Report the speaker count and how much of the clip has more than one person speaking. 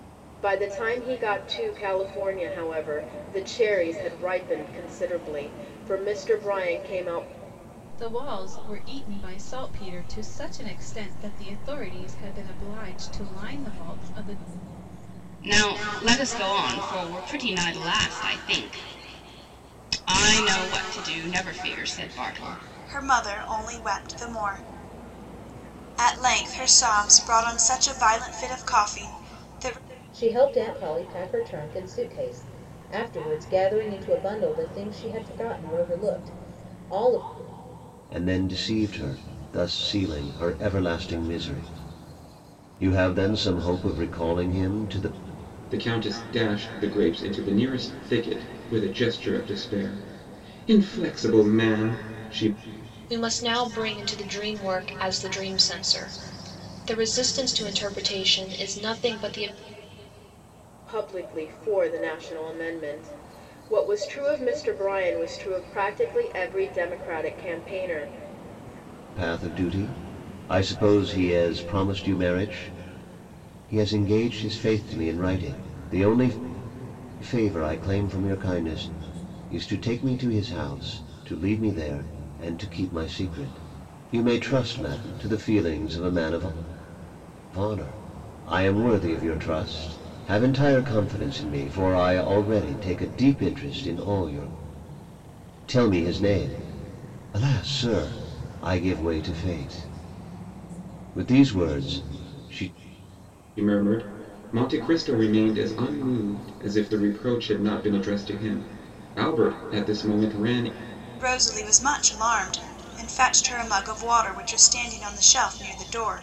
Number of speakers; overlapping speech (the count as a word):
eight, no overlap